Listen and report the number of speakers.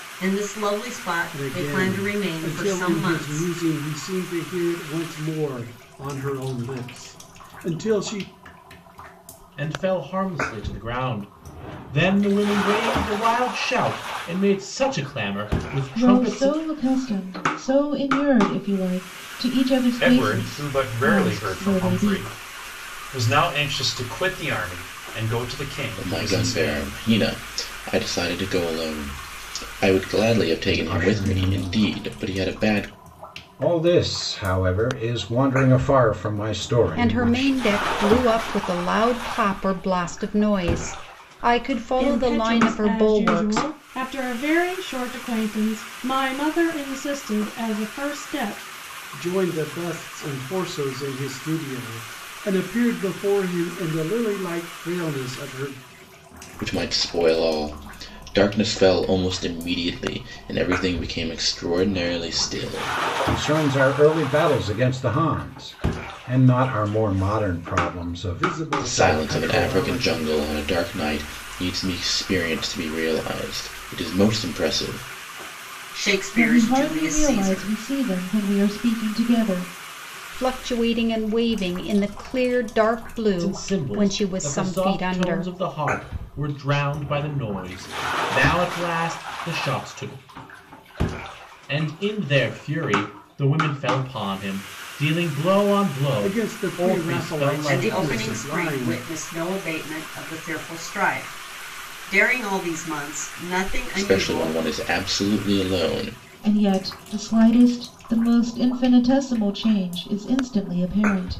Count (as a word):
nine